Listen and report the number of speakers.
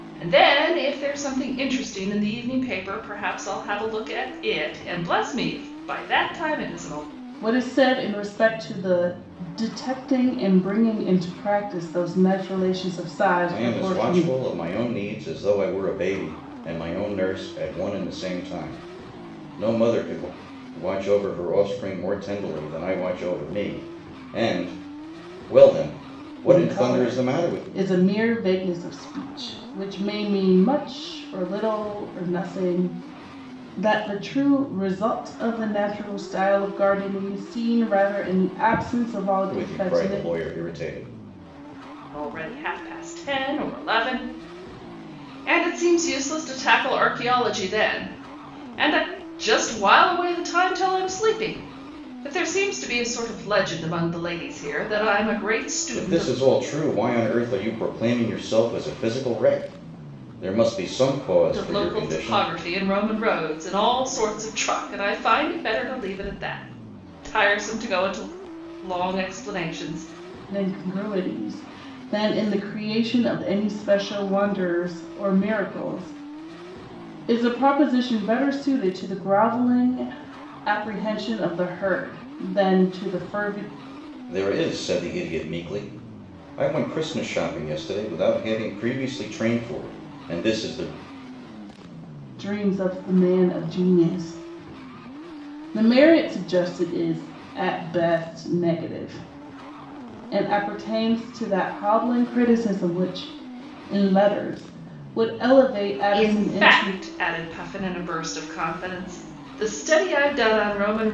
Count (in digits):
3